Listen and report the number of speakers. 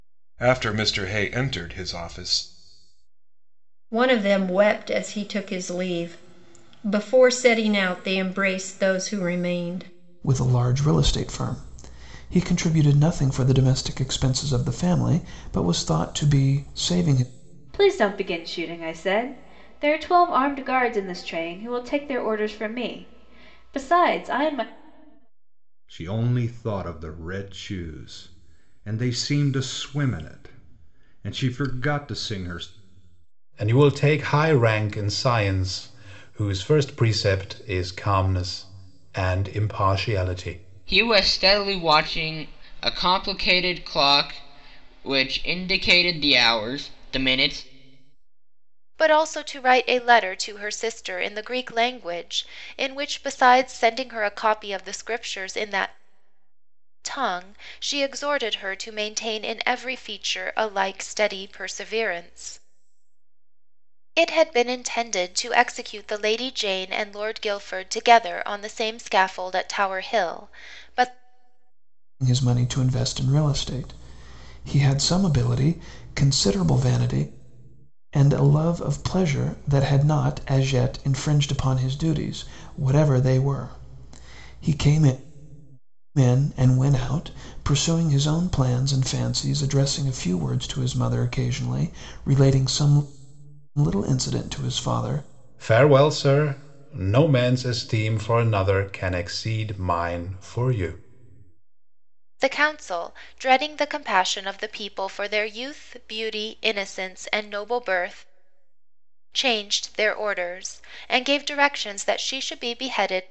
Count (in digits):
8